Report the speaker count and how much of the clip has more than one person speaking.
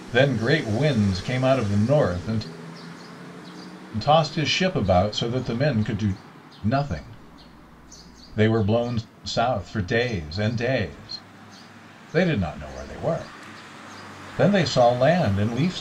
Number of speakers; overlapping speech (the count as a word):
one, no overlap